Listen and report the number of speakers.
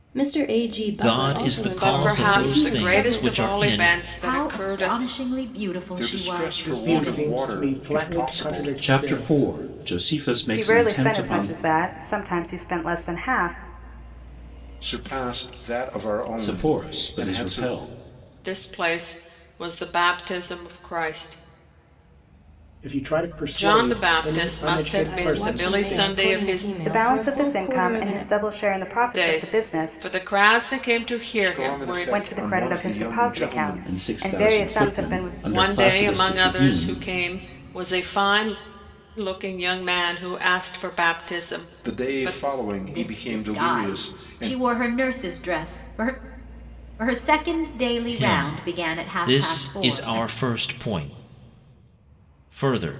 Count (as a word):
eight